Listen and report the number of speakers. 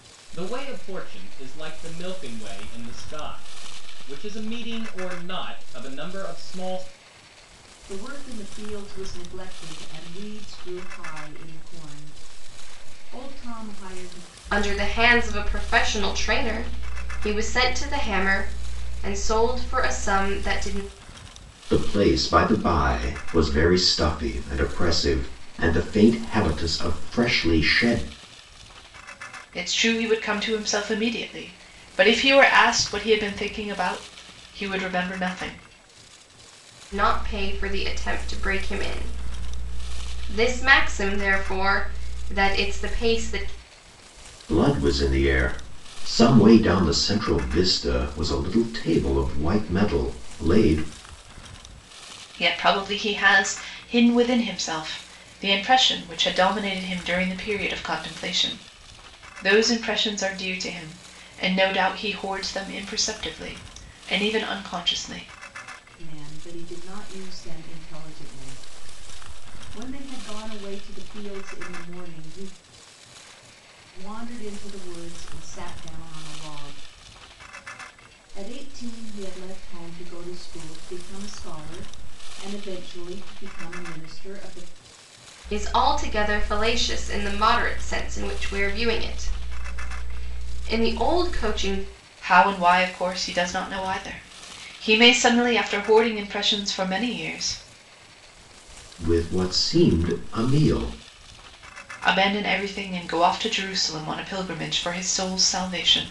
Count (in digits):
5